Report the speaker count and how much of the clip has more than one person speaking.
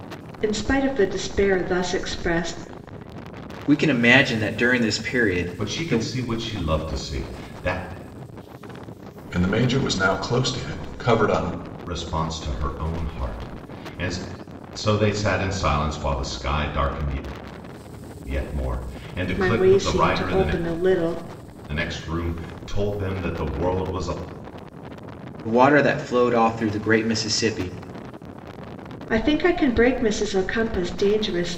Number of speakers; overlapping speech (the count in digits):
4, about 6%